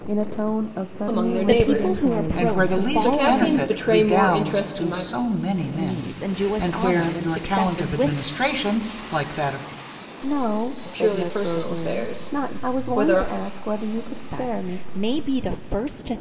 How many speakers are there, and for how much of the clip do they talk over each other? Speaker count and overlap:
four, about 58%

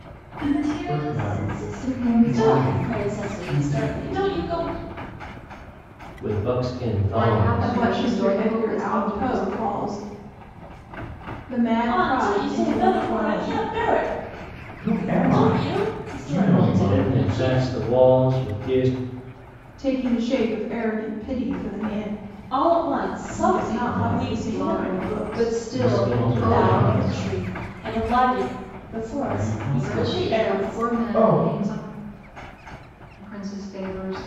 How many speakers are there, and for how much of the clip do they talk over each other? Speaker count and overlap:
seven, about 47%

